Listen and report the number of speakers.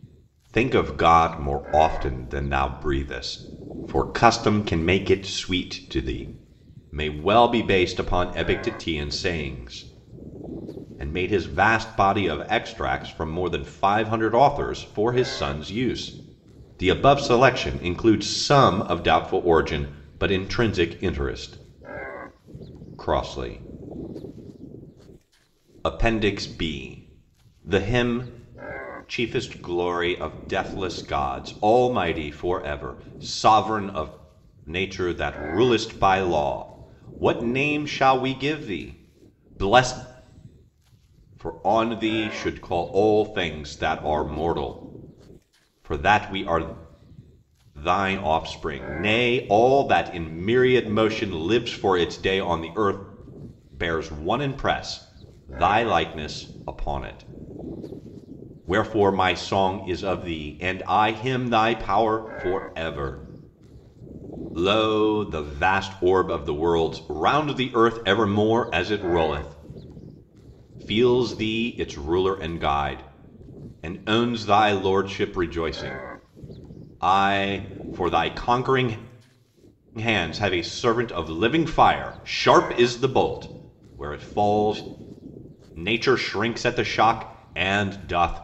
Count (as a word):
one